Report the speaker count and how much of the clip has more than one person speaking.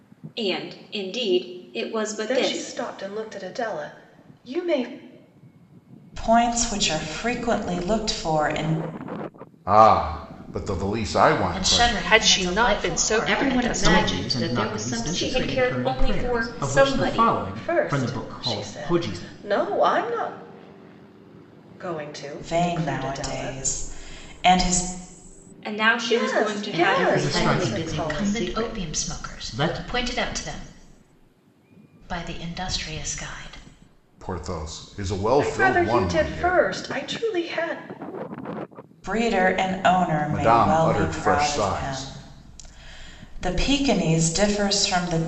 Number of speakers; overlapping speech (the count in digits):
8, about 35%